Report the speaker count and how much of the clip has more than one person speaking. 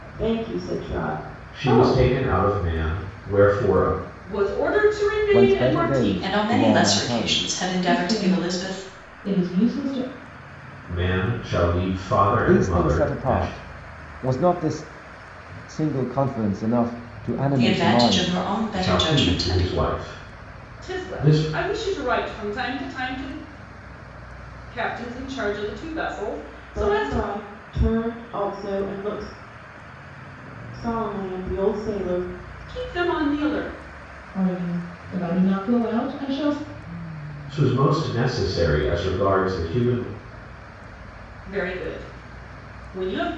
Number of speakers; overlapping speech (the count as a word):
six, about 19%